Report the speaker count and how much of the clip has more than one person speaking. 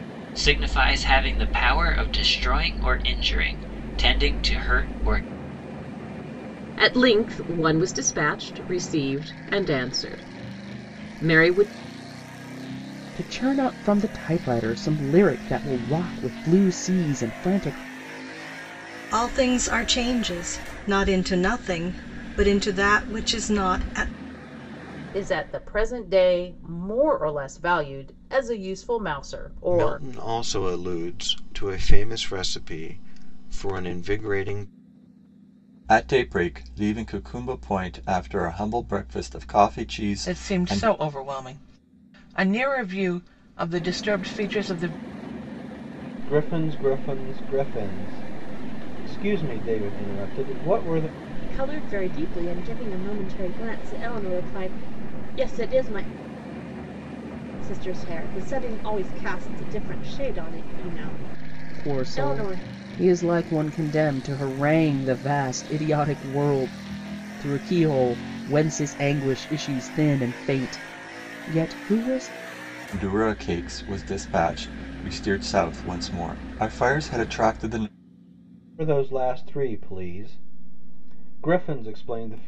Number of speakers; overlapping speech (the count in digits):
10, about 2%